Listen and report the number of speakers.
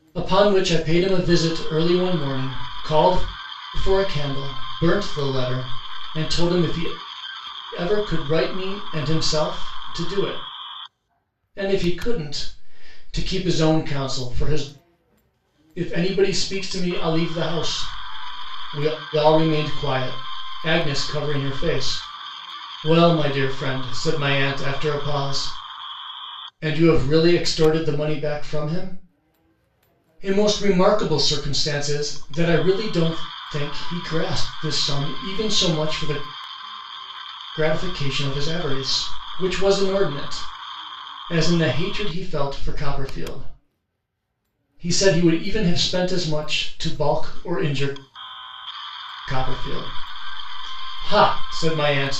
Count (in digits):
1